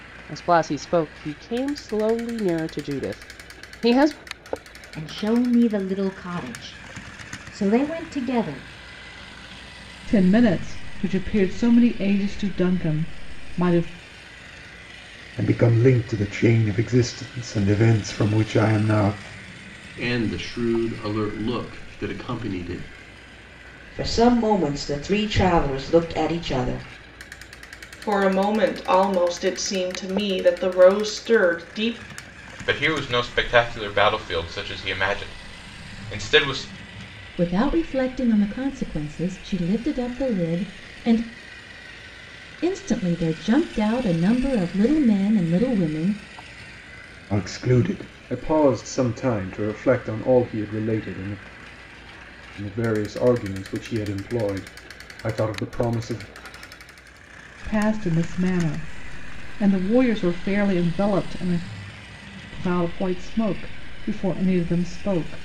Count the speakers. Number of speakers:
9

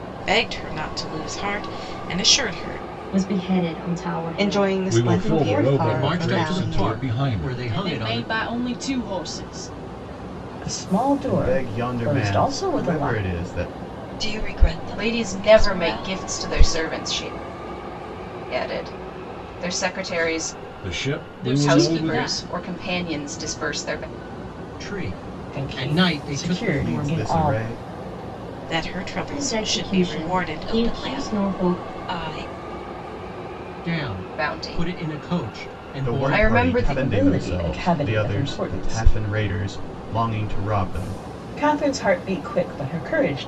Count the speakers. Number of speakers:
10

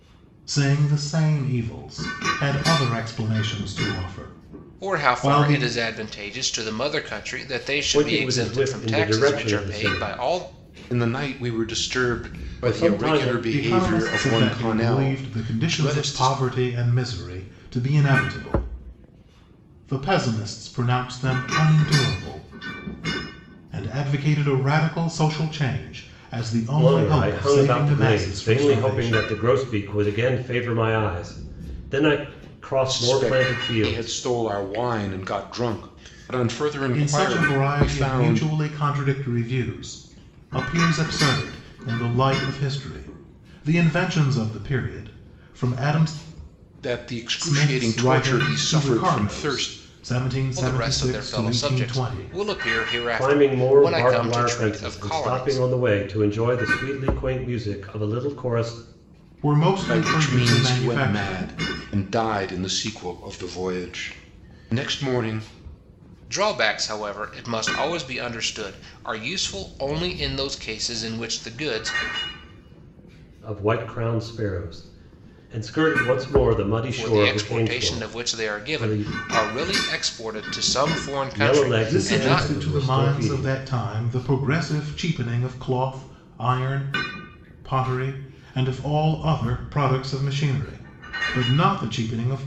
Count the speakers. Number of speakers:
4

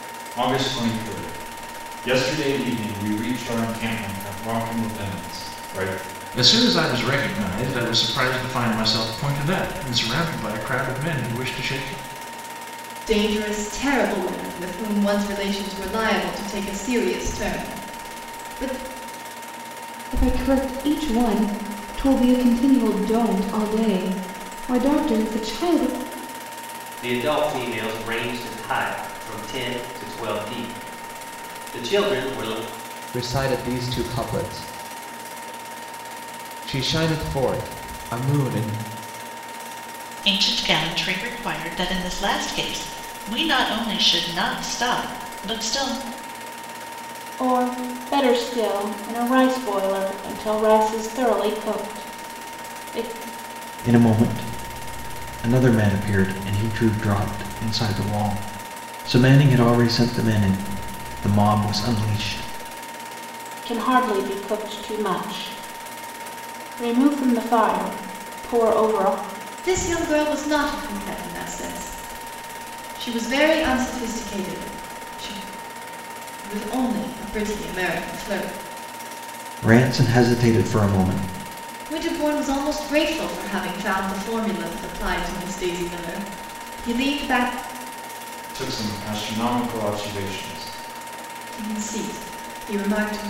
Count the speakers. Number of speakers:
9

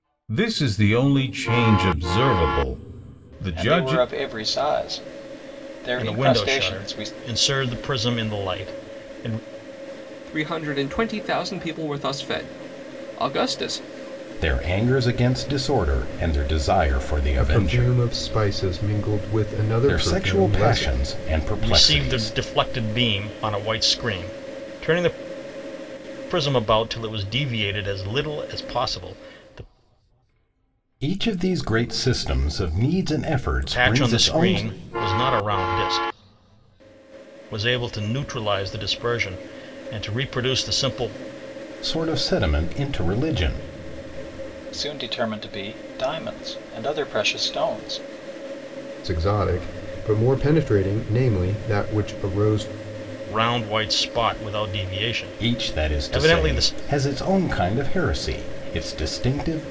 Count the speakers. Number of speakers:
6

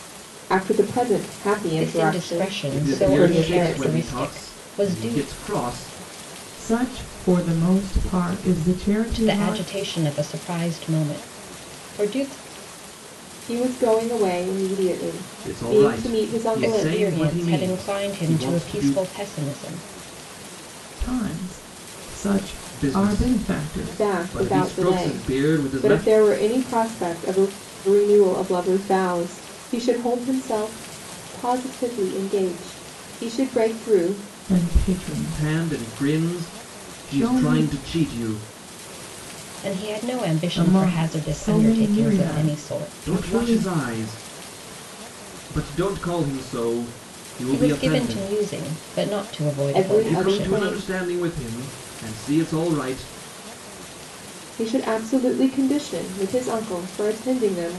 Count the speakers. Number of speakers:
4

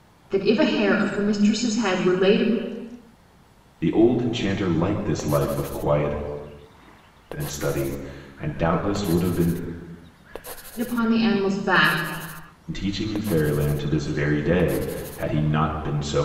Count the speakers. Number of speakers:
2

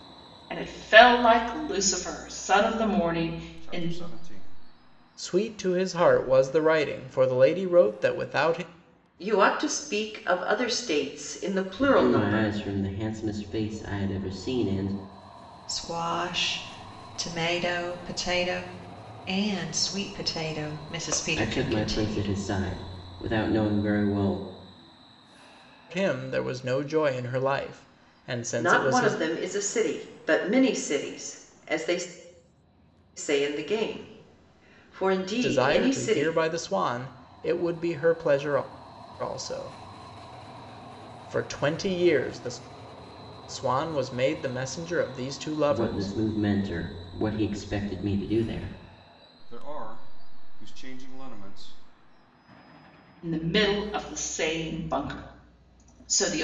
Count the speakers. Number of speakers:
6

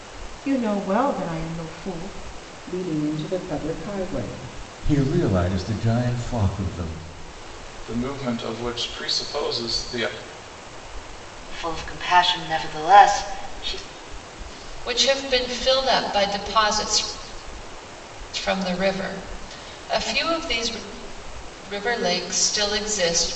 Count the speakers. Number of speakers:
6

